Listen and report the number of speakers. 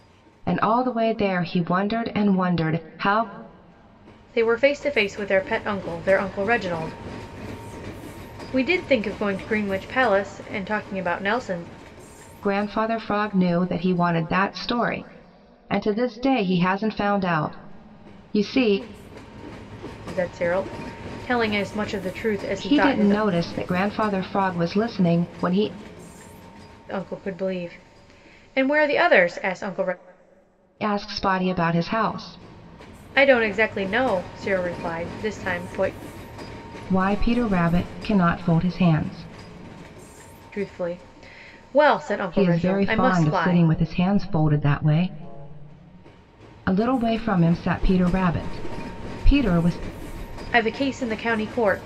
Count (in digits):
2